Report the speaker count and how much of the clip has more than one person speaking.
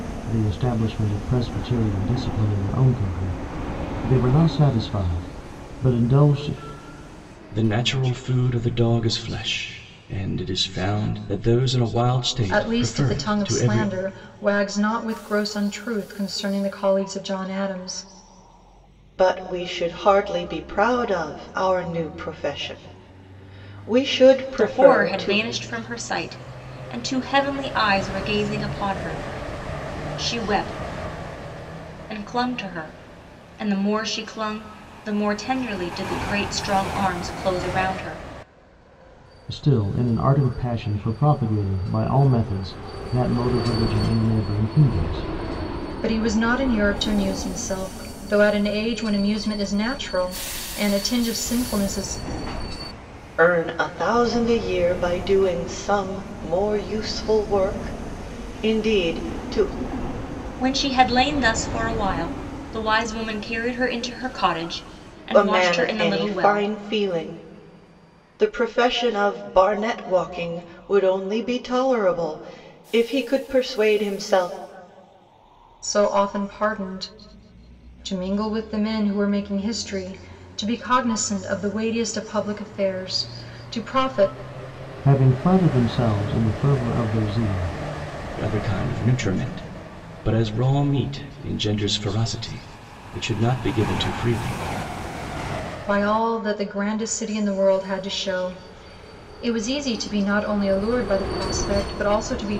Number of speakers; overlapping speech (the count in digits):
5, about 4%